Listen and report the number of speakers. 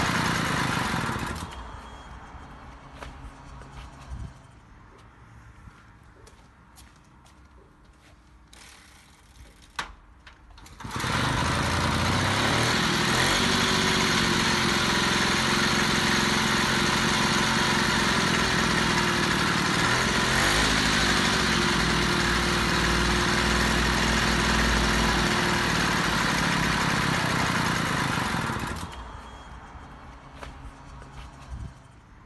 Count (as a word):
zero